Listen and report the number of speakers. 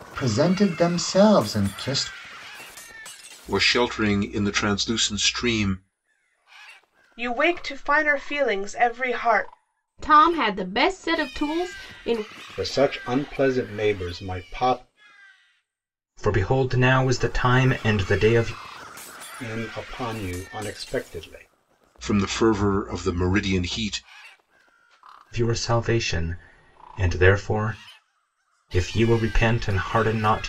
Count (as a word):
six